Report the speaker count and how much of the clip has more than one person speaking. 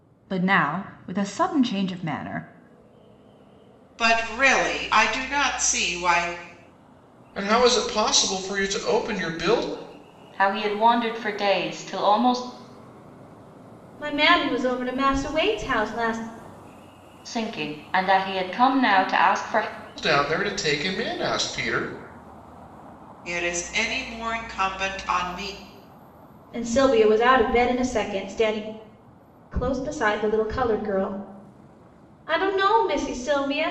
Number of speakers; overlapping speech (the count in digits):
5, no overlap